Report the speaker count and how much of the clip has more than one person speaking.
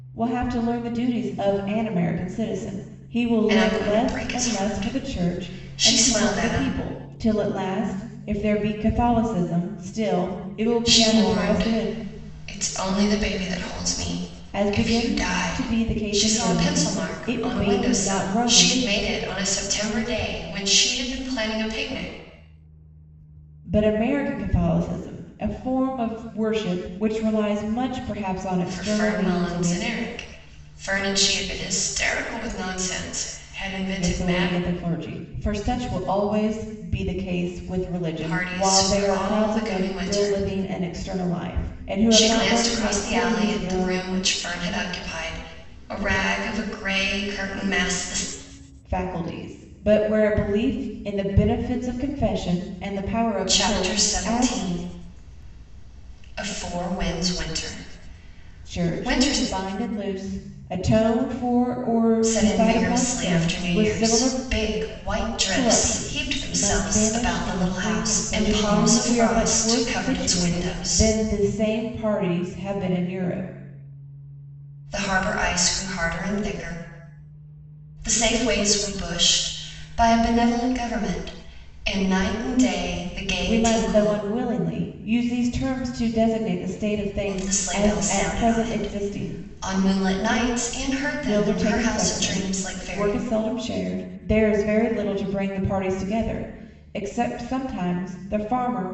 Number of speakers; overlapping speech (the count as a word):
two, about 29%